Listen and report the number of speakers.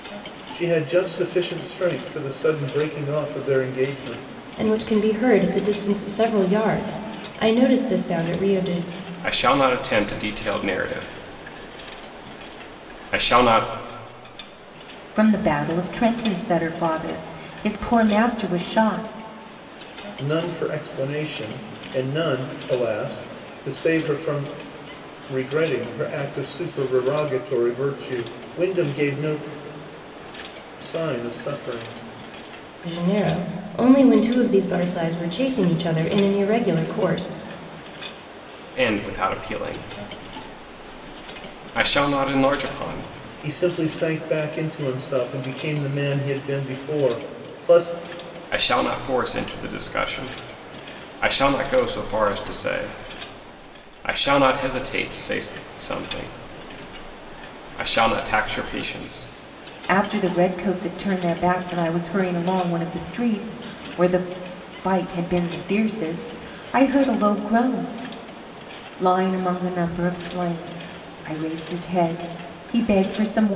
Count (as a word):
four